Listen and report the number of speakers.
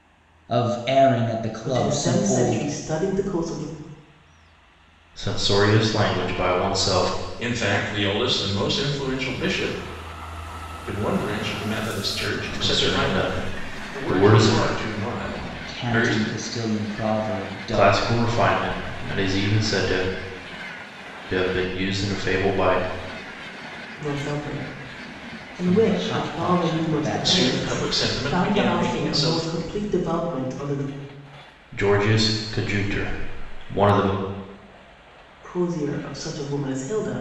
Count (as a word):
four